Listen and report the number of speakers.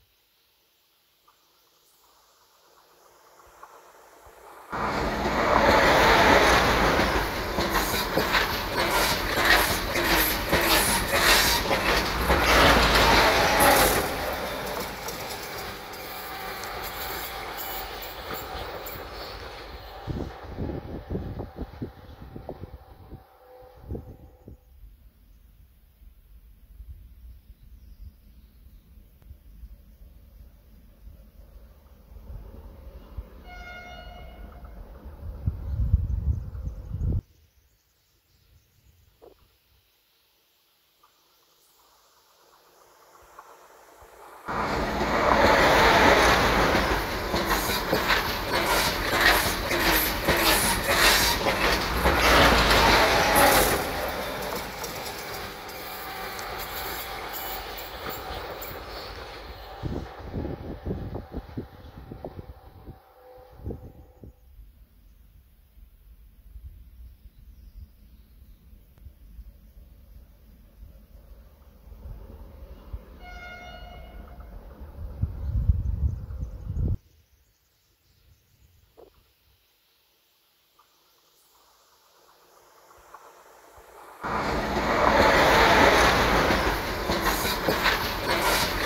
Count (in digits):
0